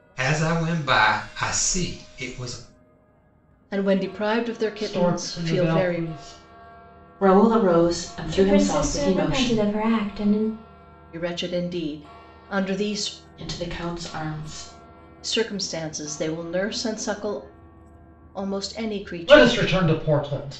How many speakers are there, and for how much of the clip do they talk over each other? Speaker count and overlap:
5, about 15%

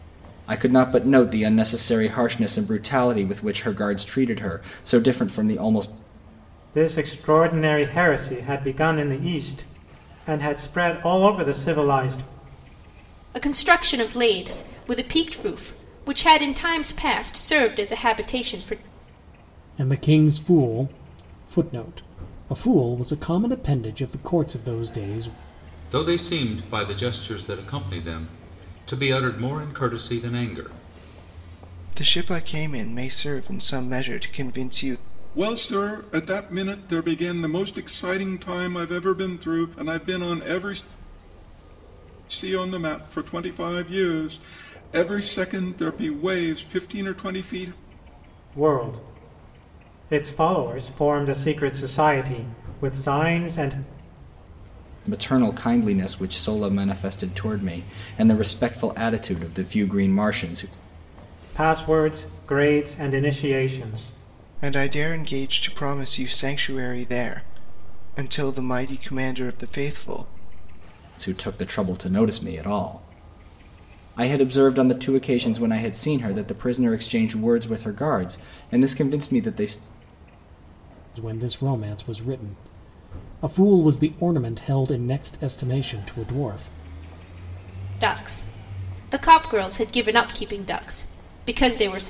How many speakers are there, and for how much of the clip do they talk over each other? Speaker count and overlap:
7, no overlap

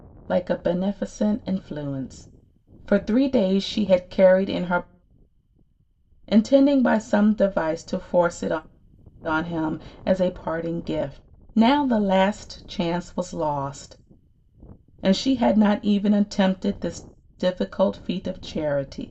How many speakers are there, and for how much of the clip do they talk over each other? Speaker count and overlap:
1, no overlap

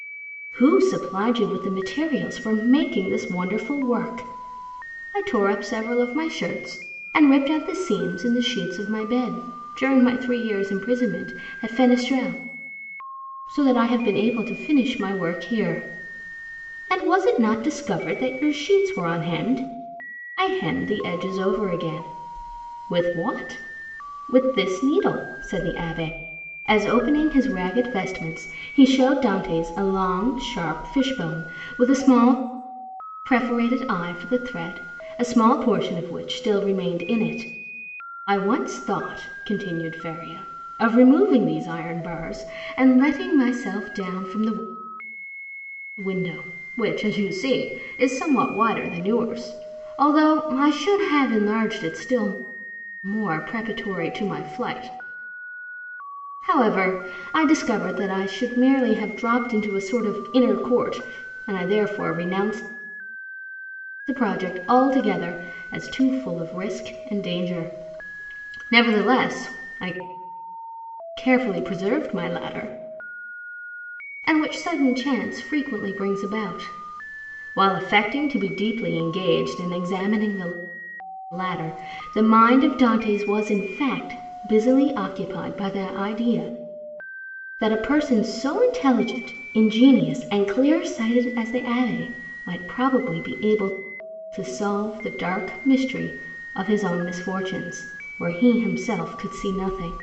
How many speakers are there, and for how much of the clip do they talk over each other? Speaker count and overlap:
1, no overlap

